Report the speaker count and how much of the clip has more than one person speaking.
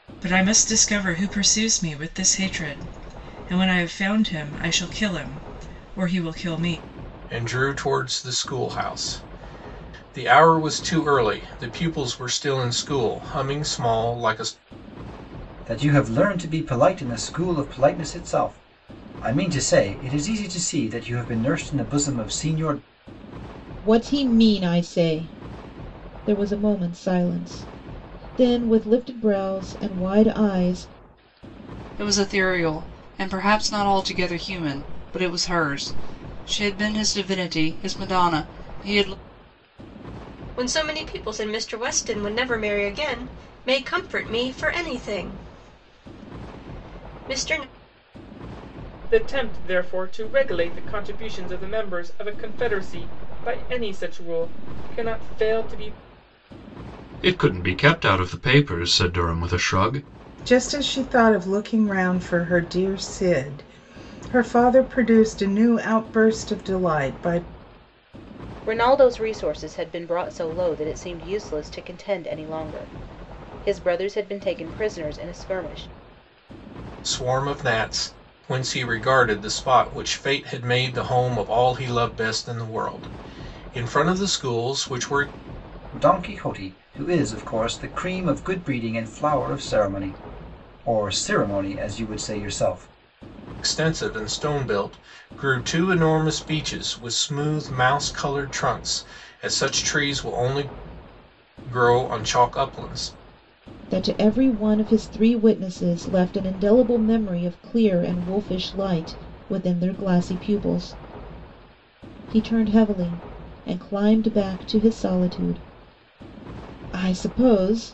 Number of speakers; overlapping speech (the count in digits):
10, no overlap